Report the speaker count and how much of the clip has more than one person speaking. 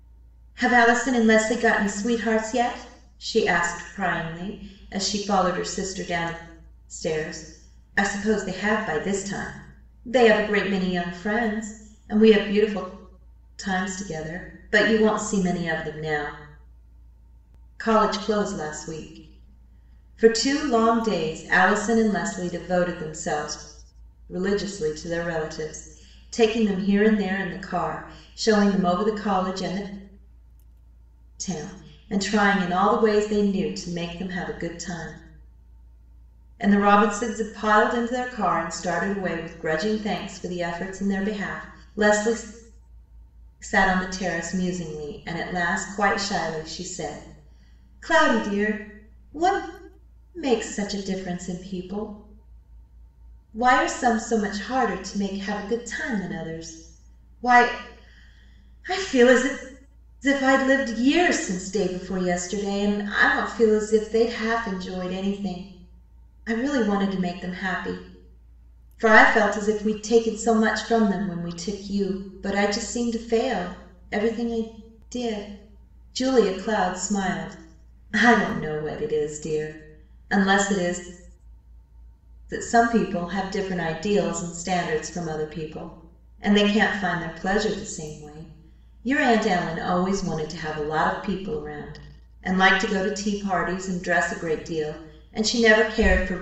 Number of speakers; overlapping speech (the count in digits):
1, no overlap